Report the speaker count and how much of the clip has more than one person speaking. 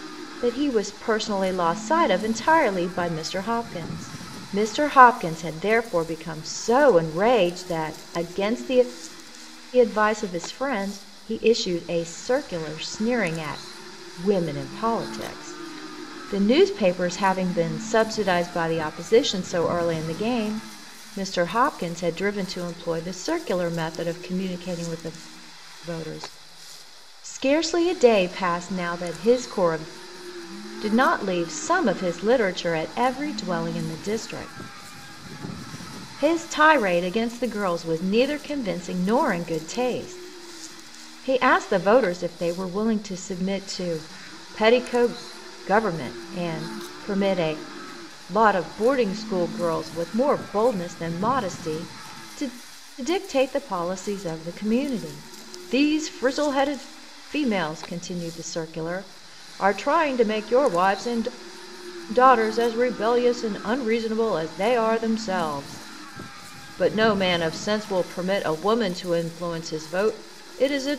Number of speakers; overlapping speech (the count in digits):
1, no overlap